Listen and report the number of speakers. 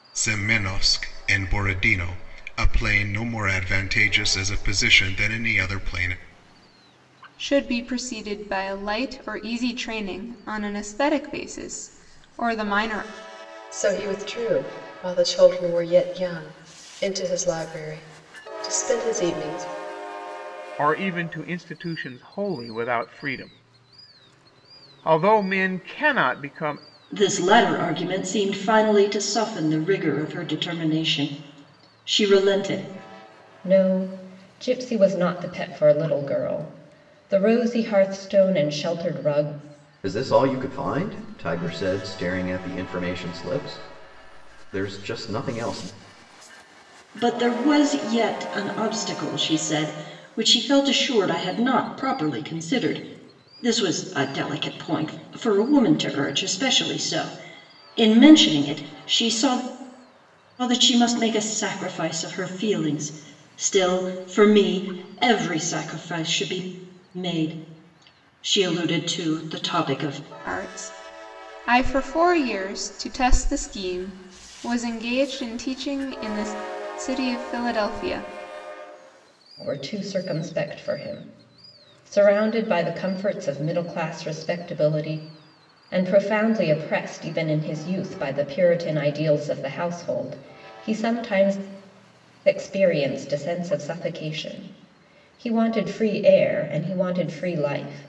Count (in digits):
7